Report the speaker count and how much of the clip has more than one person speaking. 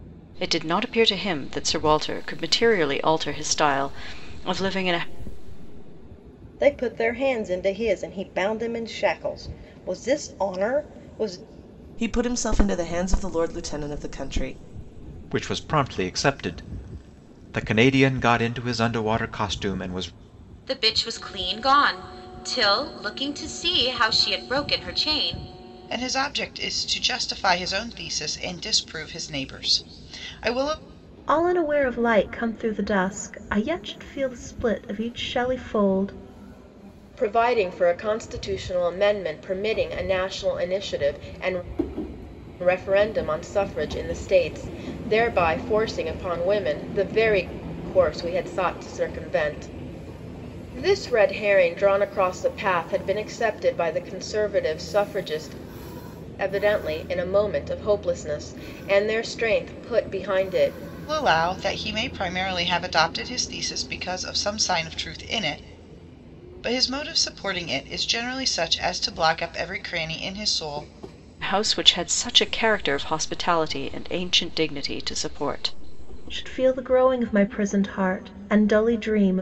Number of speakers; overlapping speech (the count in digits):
8, no overlap